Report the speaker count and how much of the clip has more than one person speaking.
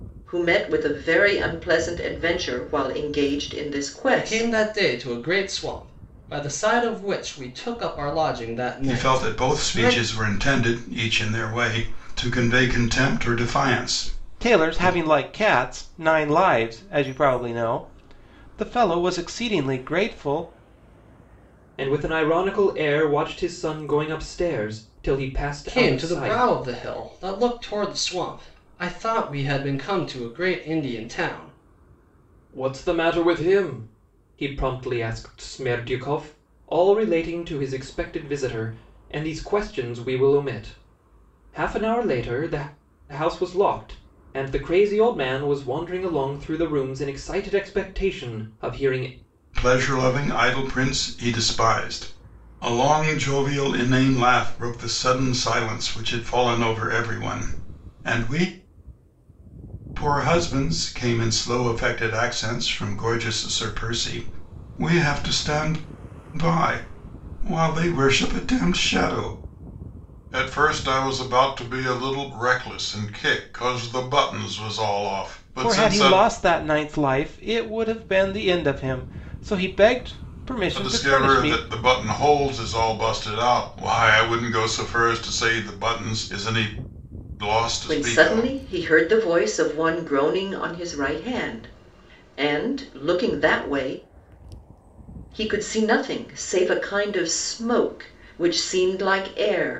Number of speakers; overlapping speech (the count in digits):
5, about 6%